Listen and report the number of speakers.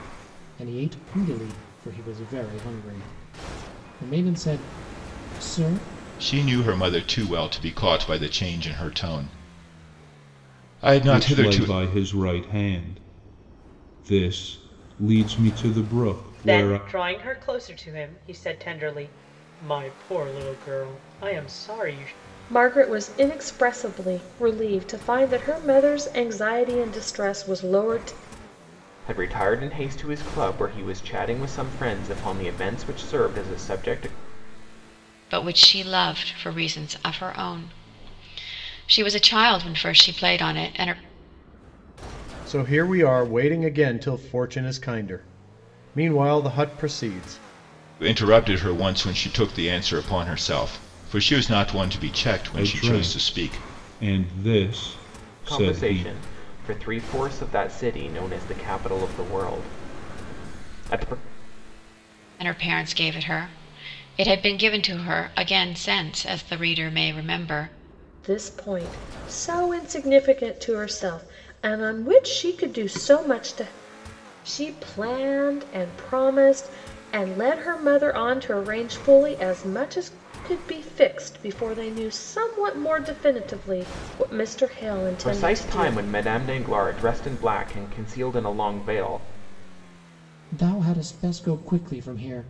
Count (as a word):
eight